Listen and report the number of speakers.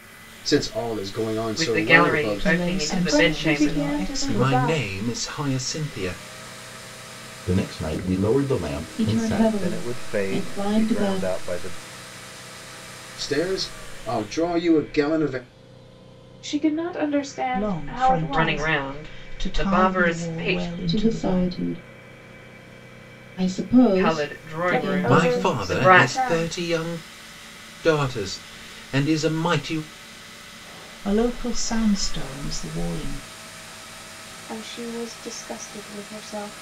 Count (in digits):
8